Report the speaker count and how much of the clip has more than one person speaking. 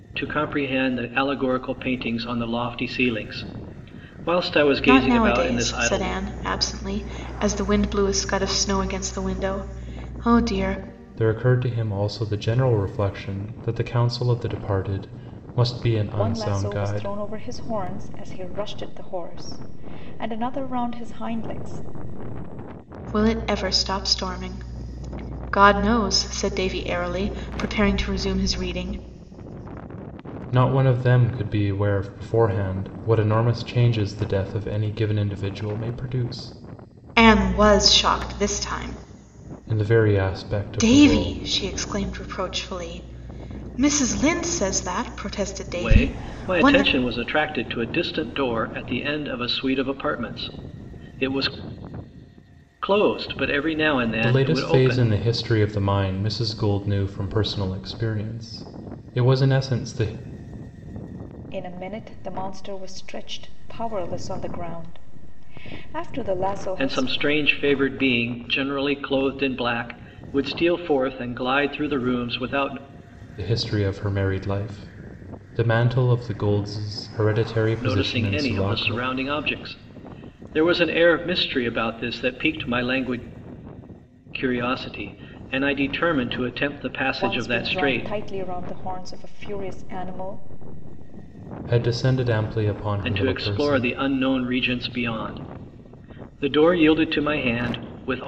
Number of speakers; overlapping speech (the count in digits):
4, about 9%